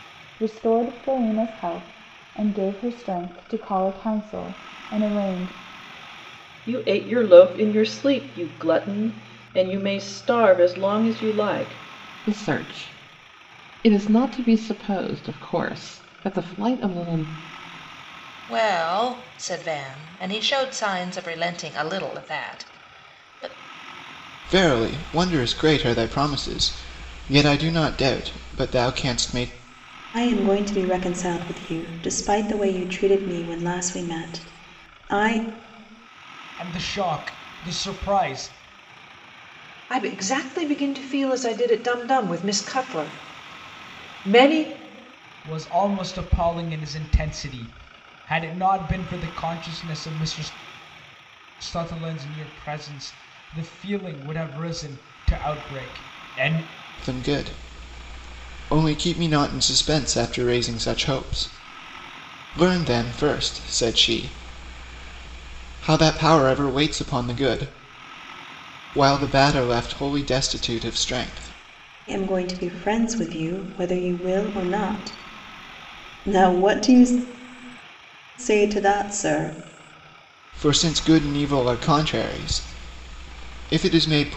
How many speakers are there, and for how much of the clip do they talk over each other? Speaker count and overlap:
8, no overlap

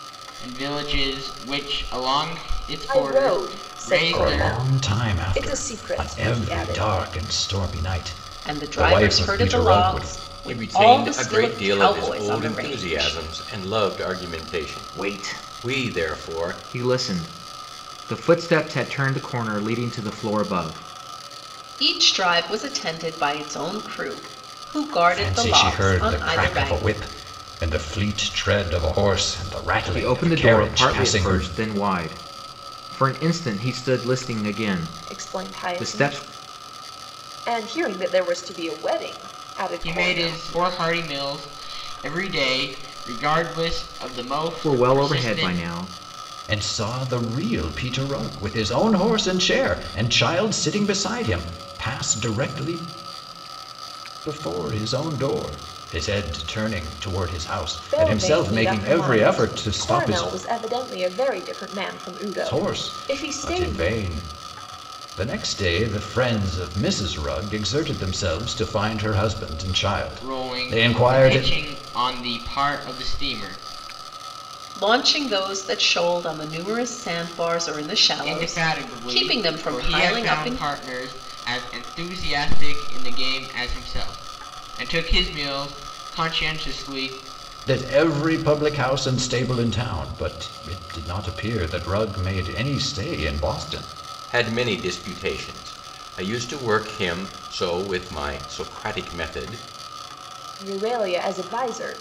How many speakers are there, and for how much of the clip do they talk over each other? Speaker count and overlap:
6, about 24%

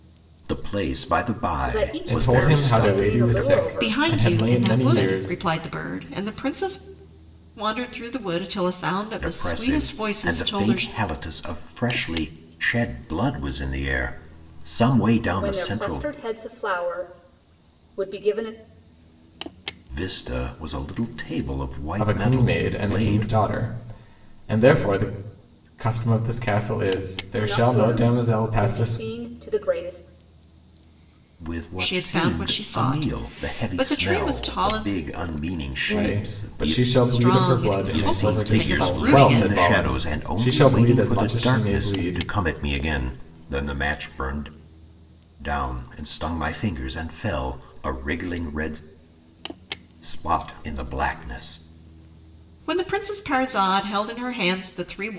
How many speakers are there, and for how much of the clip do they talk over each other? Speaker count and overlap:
4, about 34%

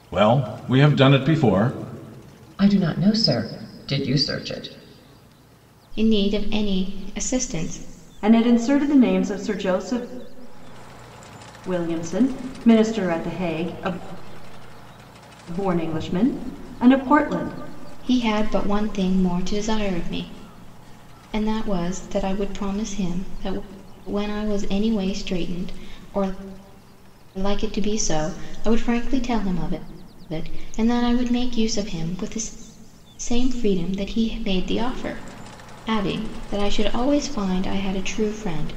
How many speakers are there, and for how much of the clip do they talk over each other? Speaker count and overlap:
4, no overlap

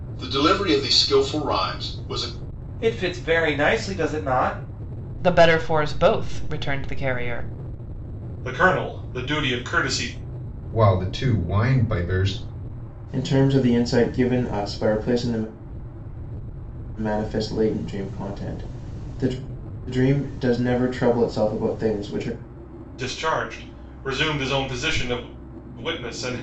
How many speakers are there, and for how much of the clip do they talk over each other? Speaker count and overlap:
6, no overlap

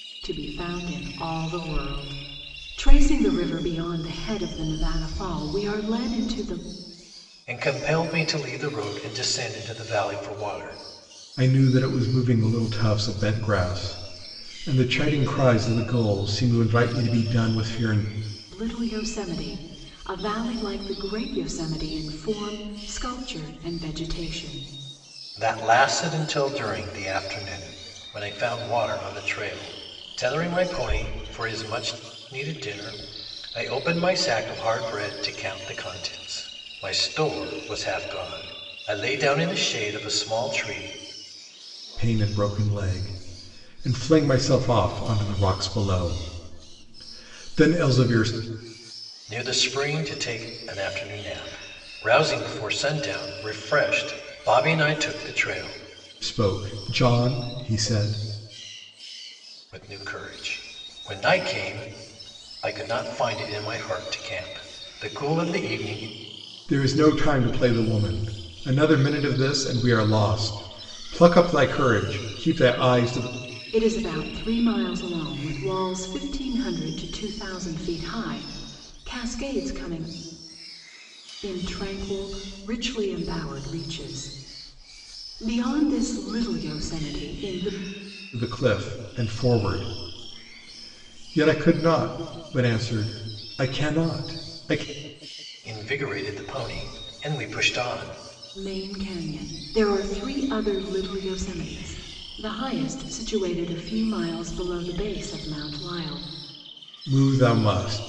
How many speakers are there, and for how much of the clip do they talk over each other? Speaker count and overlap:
3, no overlap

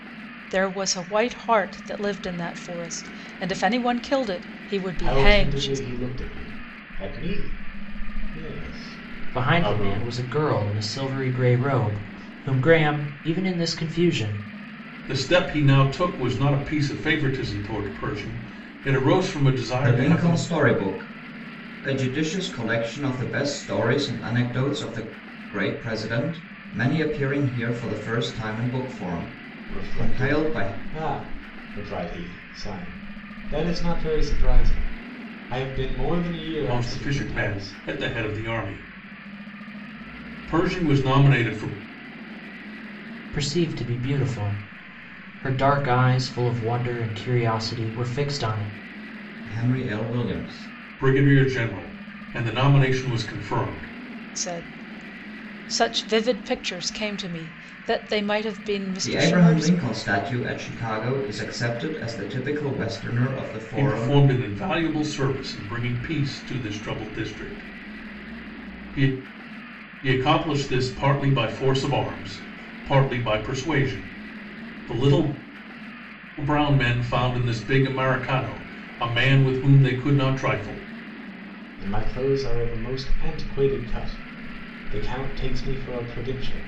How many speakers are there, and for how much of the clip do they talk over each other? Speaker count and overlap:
5, about 7%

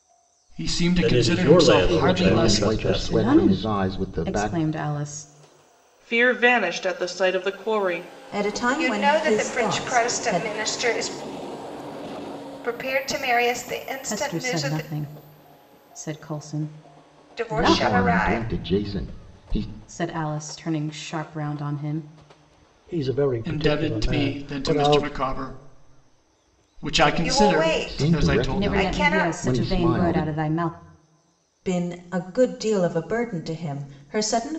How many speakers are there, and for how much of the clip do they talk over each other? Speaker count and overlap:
8, about 36%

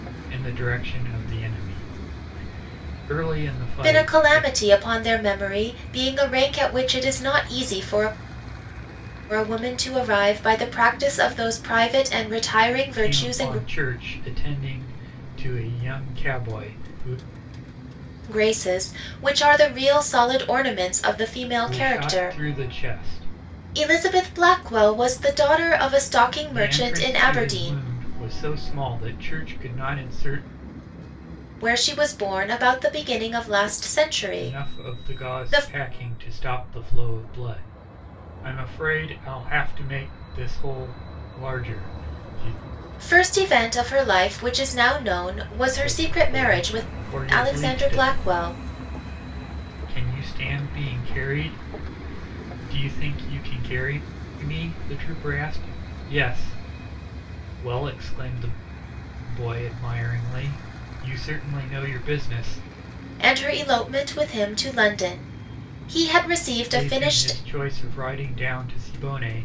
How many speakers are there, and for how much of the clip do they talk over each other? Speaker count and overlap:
2, about 11%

